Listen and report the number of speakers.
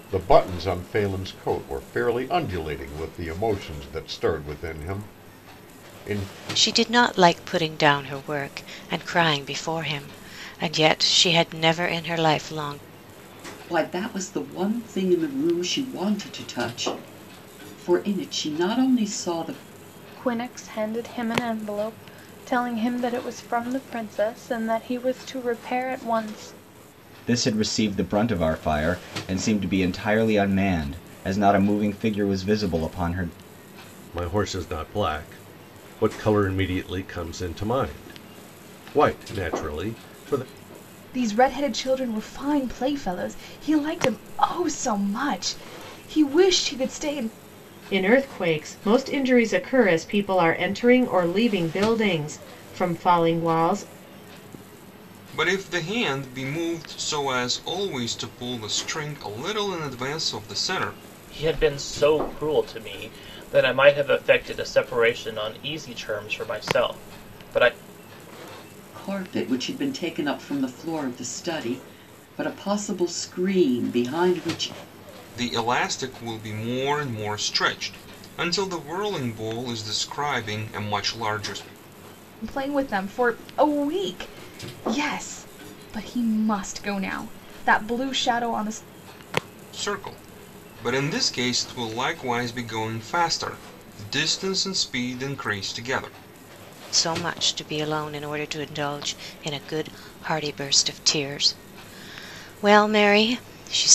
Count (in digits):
10